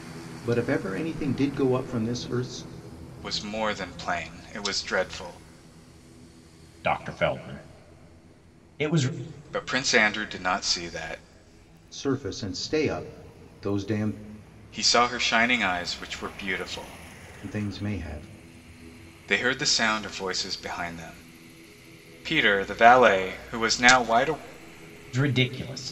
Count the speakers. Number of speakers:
3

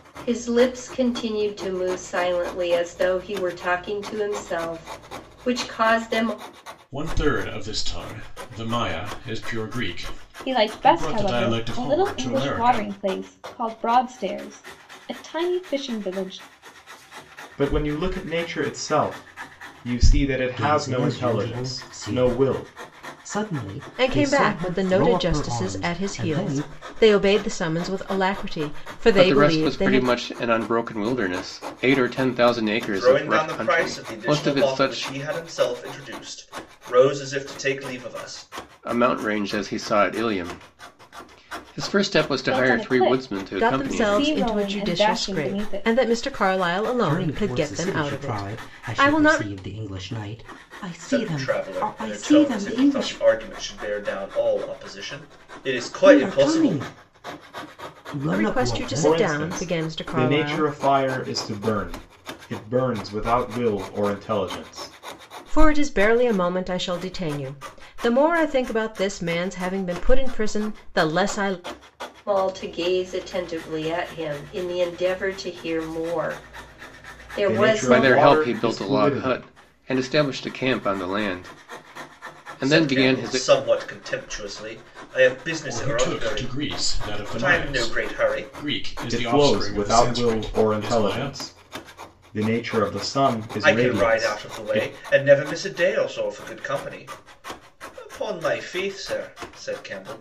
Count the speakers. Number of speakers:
8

